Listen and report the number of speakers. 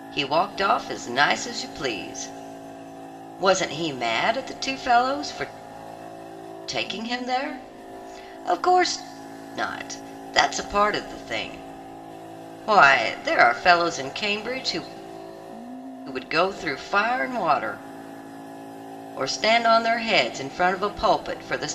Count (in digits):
1